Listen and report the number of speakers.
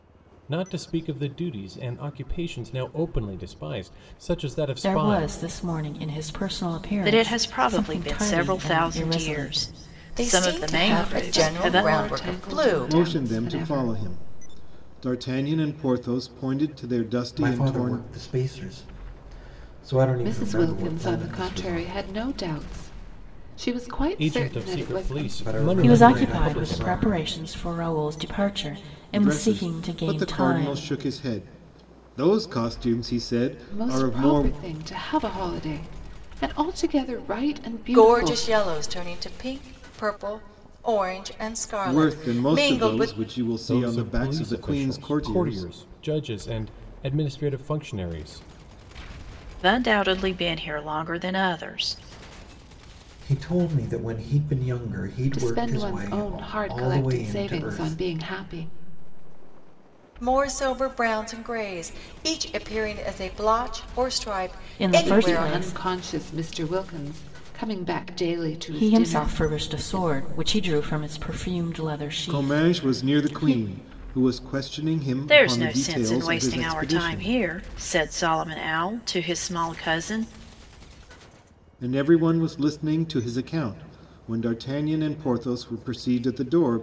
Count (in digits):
7